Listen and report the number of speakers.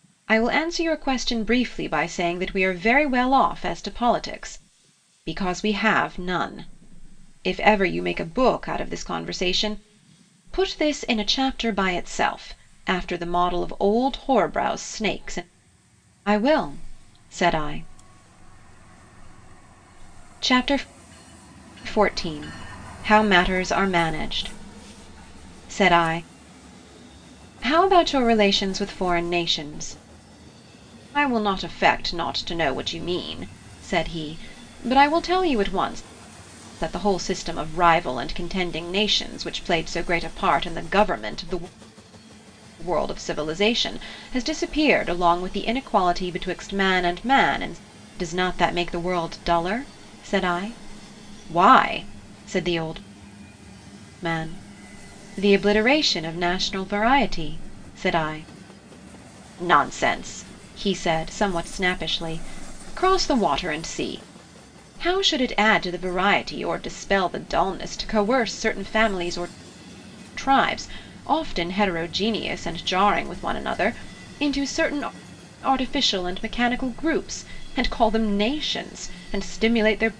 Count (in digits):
1